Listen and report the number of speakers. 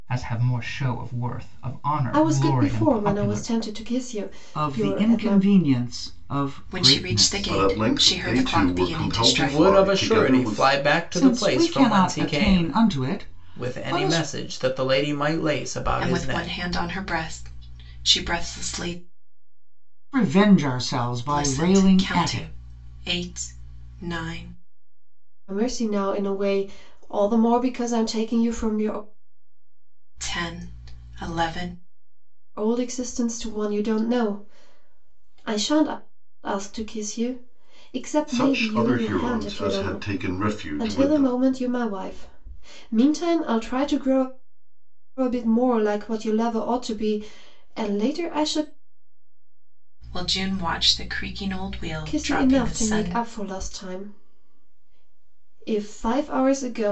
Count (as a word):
six